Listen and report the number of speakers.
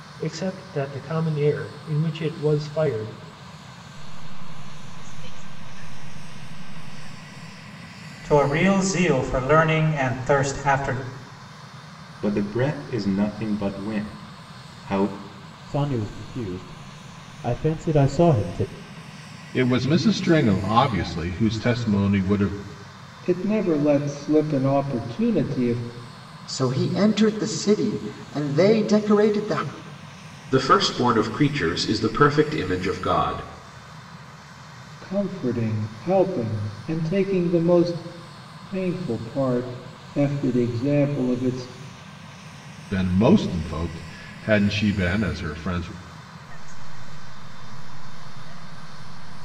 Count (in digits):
9